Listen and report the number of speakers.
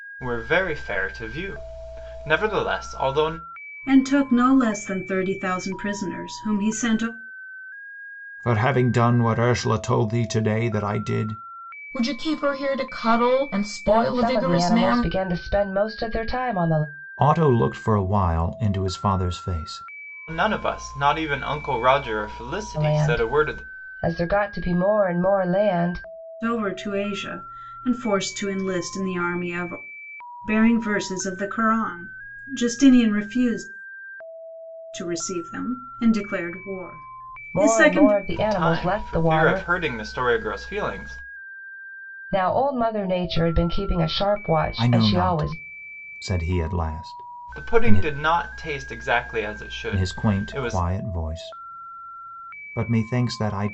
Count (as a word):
five